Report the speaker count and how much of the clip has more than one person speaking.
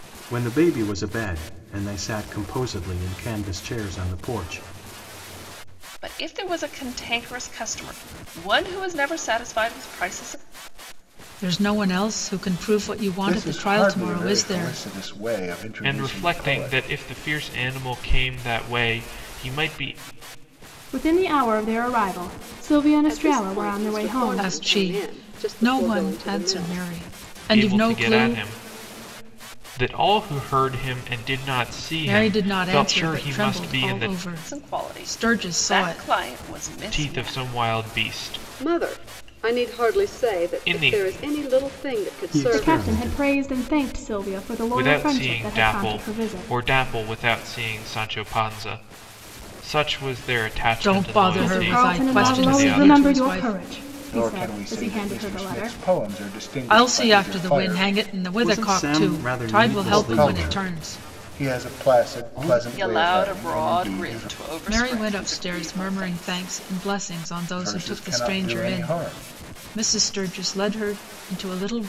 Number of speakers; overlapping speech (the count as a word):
seven, about 46%